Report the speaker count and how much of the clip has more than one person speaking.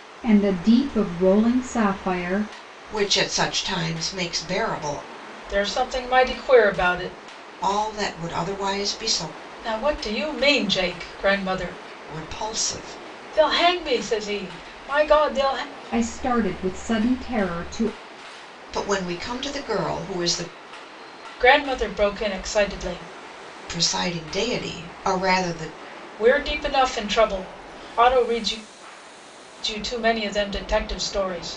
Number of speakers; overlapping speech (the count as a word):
three, no overlap